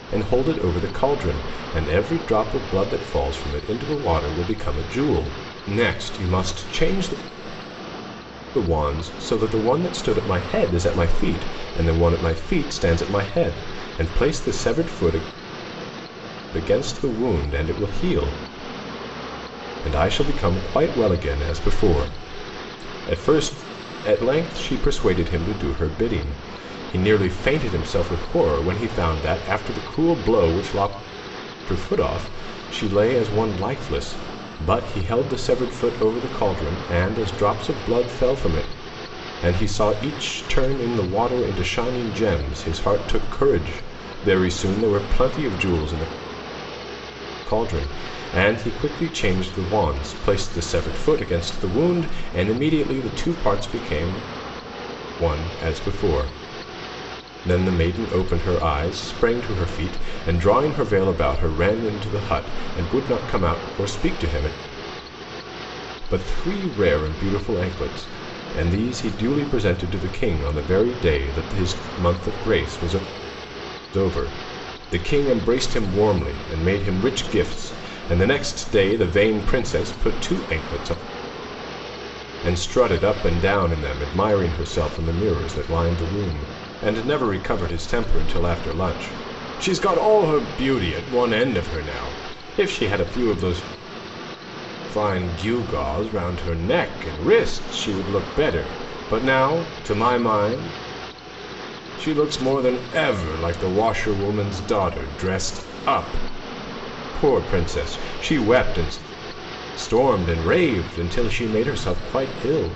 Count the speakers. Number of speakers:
one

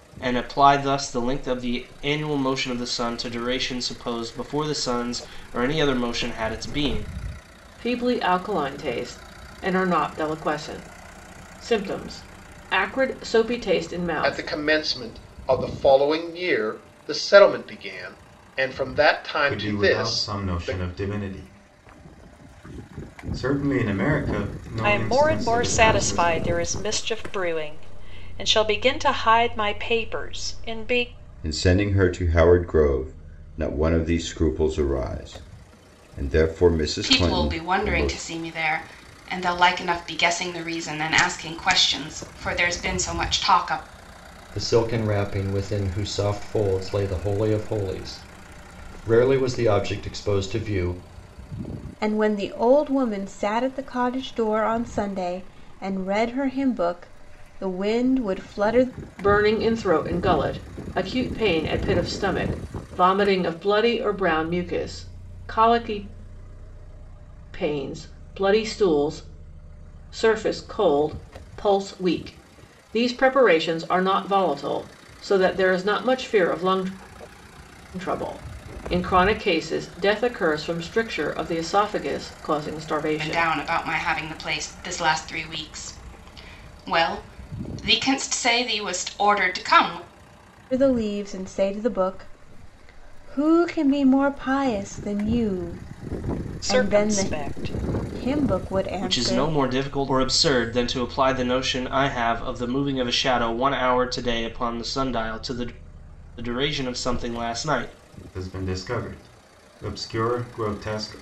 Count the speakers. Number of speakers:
nine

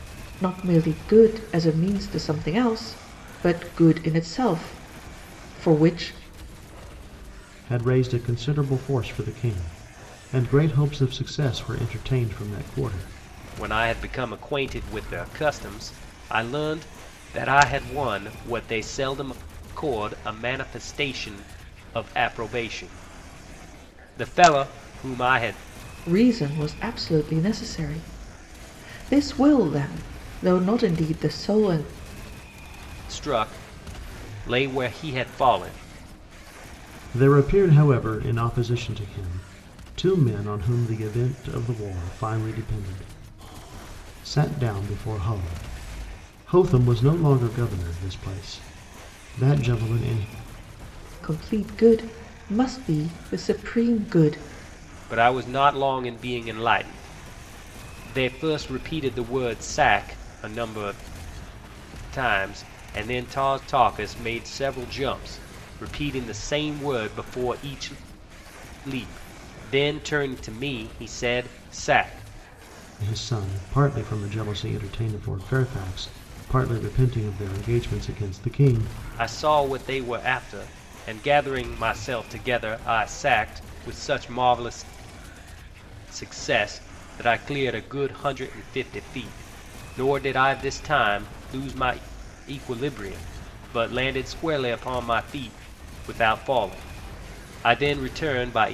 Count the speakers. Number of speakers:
three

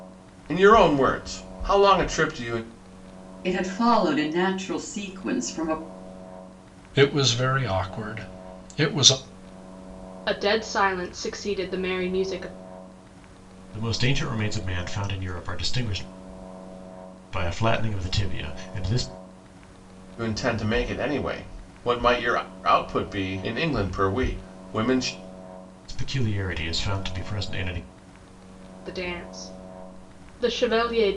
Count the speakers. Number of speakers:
five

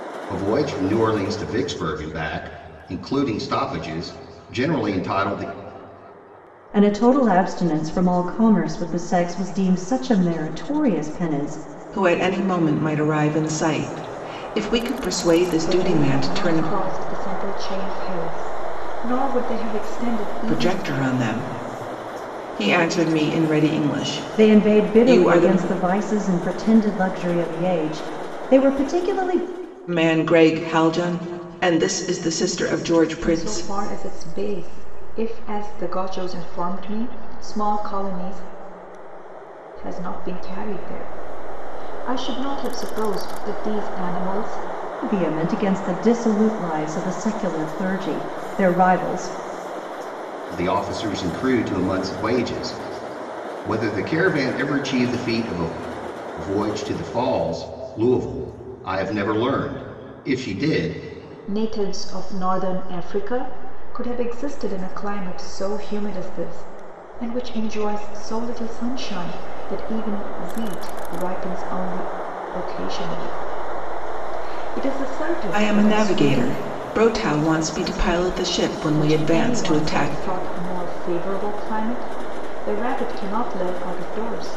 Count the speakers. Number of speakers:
four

